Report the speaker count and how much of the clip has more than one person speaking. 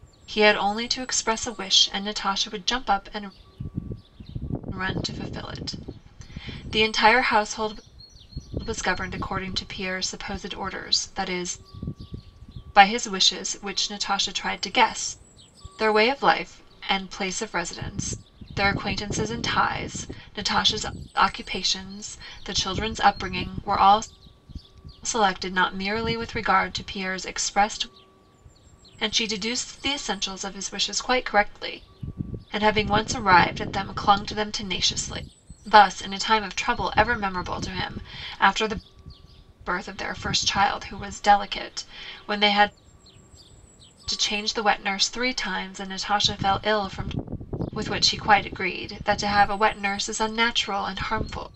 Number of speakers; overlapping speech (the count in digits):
1, no overlap